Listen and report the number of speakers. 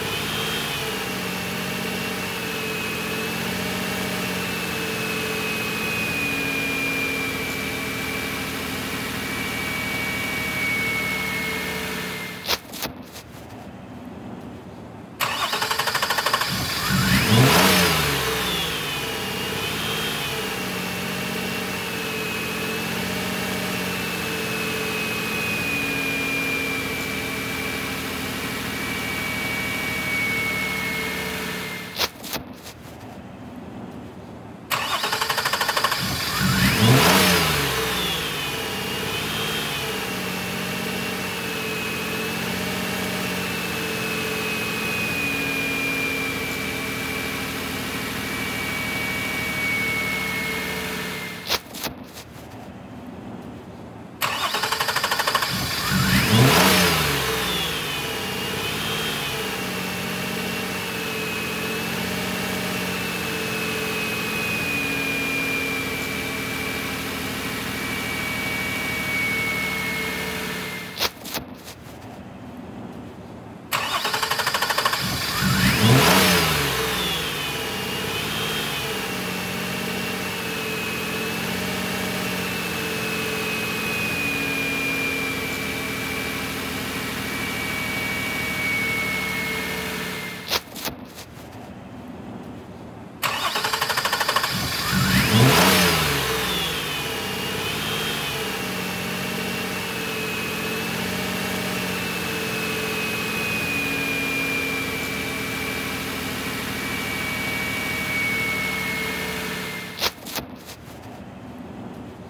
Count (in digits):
0